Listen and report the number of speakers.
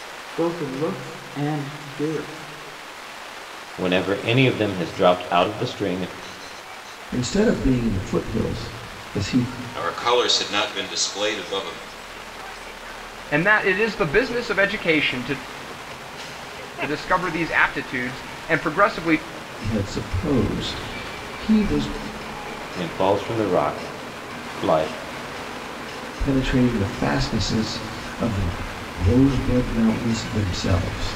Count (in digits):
5